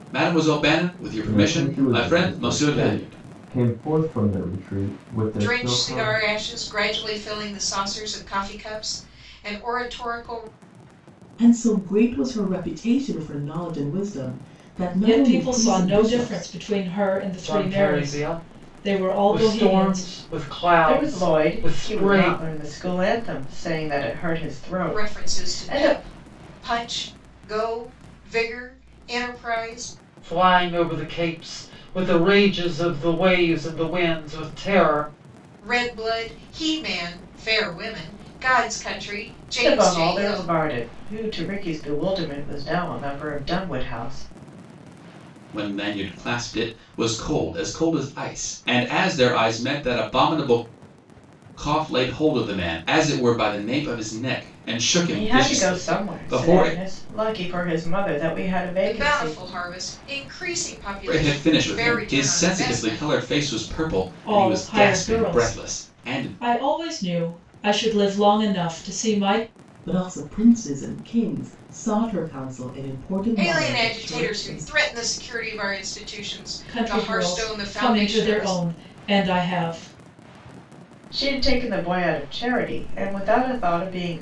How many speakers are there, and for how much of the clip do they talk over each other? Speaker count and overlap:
seven, about 24%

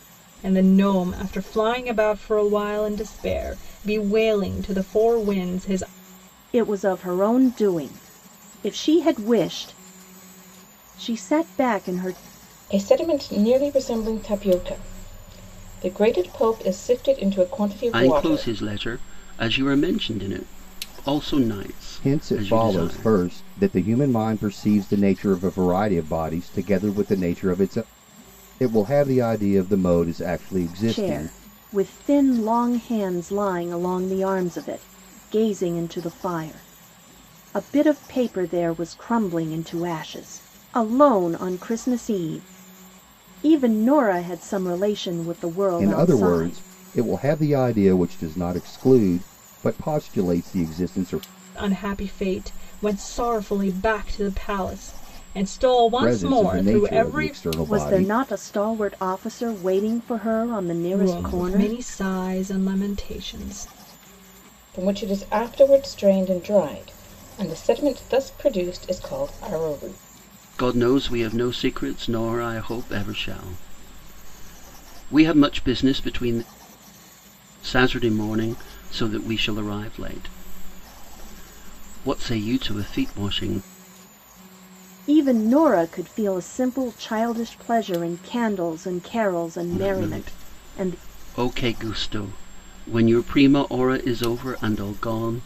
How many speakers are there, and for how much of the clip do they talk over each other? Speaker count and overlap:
five, about 8%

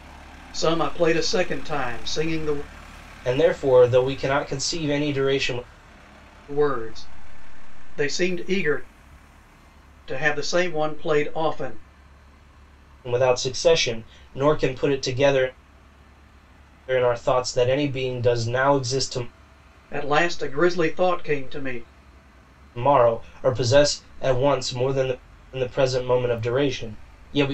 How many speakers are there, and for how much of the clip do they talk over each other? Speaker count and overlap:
two, no overlap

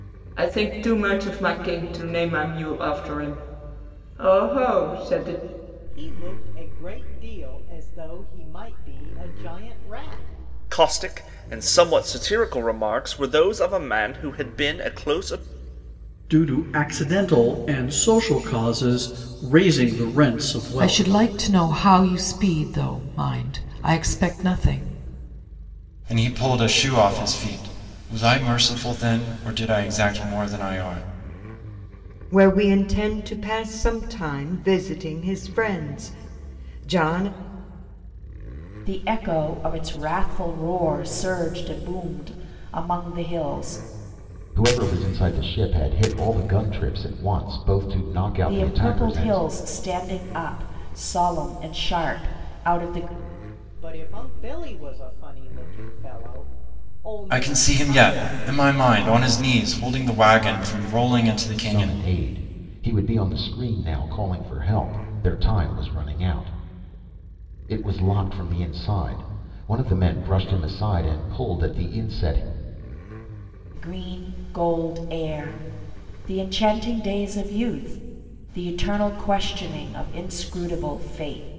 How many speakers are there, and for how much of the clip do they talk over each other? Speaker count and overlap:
nine, about 4%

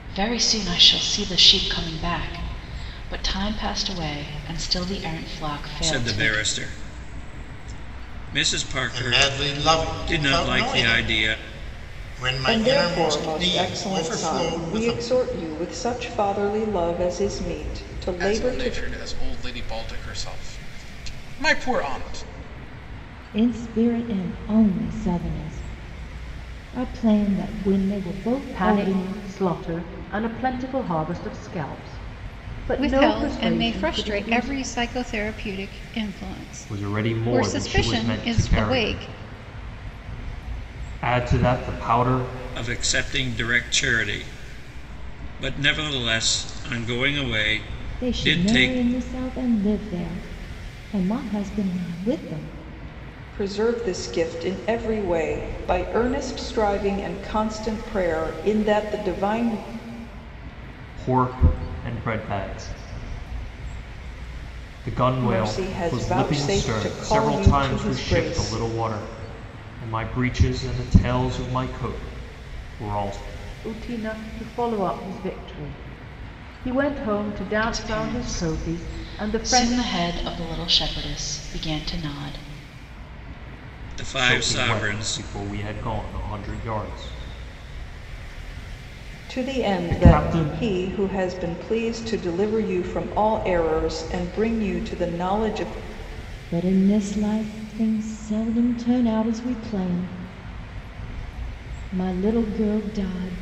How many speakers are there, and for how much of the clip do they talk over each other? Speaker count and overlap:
nine, about 20%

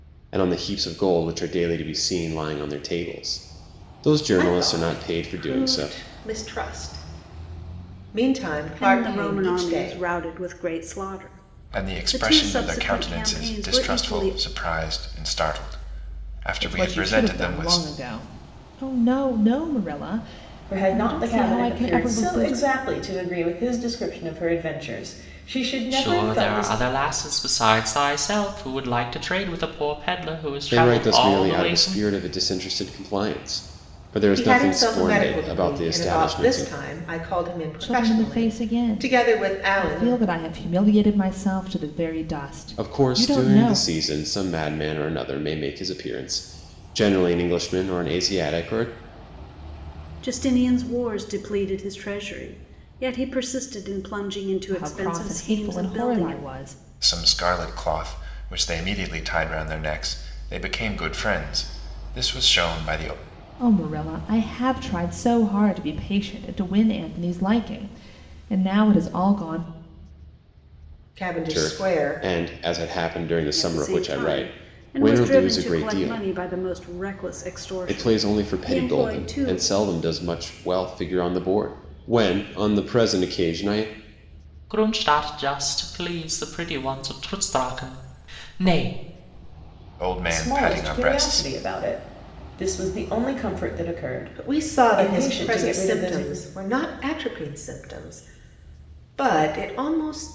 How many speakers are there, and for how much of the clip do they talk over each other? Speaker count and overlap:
seven, about 27%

